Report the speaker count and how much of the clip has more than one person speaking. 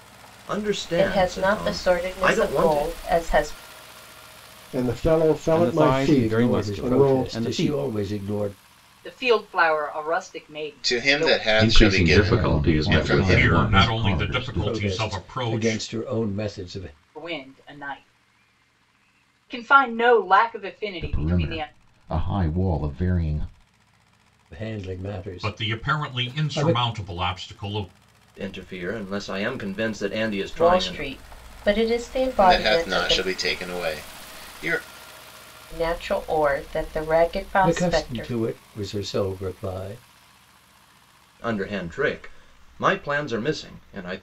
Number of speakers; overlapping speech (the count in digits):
10, about 30%